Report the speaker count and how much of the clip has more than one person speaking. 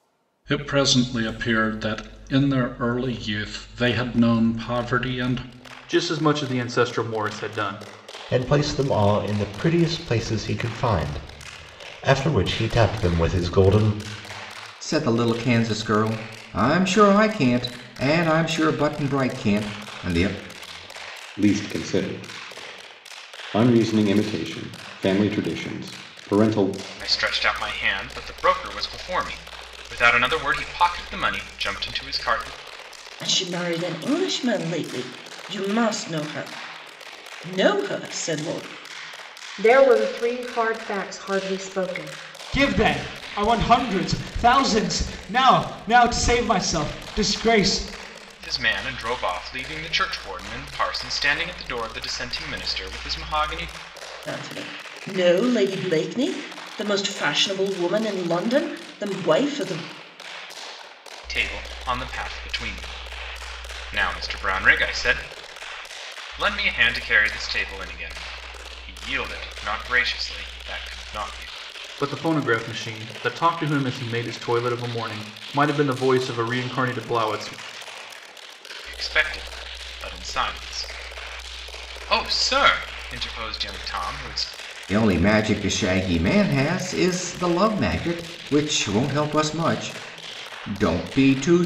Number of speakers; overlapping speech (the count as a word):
nine, no overlap